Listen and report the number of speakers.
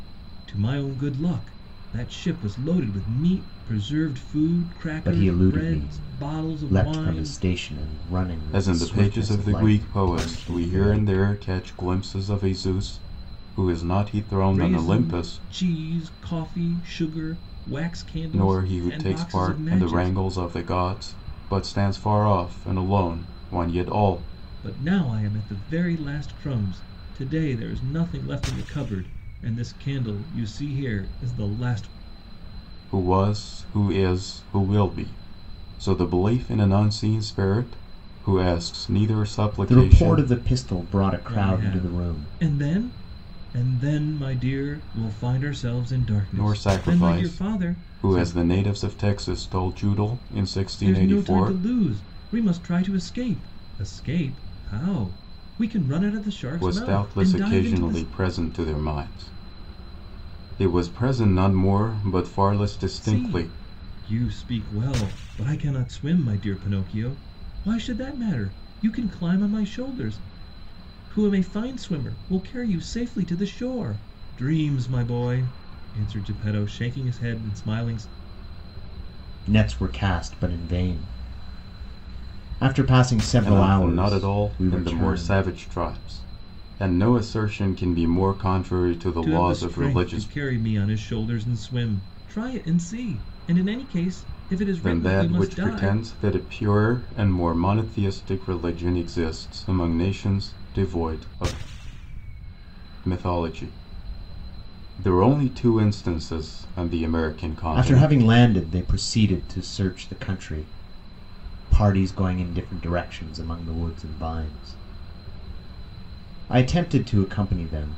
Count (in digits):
3